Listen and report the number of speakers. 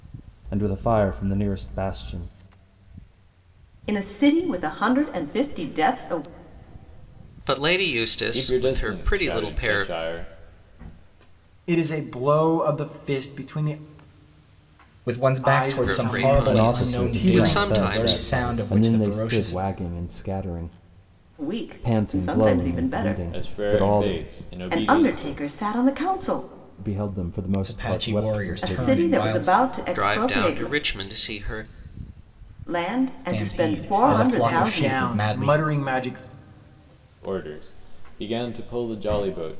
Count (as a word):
six